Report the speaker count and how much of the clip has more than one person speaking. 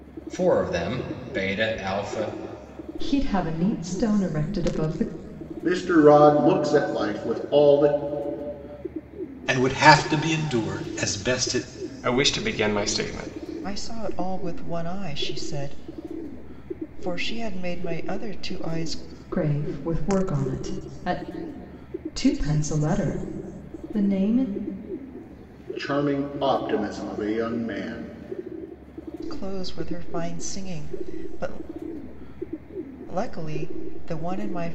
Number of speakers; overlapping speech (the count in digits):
6, no overlap